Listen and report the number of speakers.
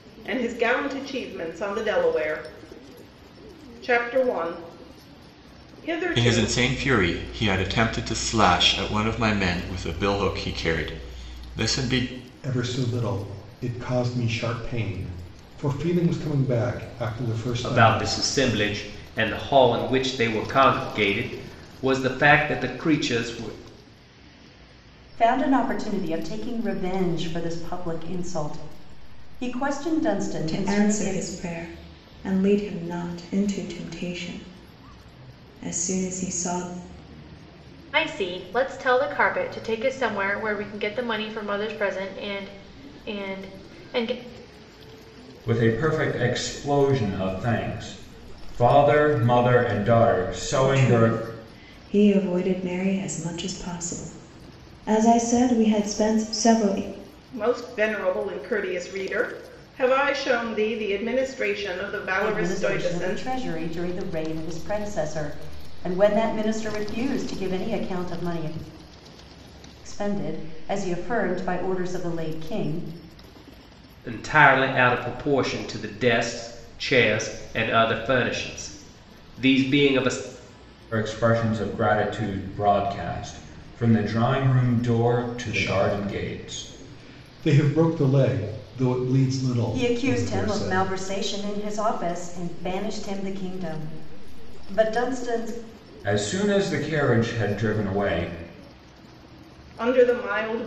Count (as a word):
eight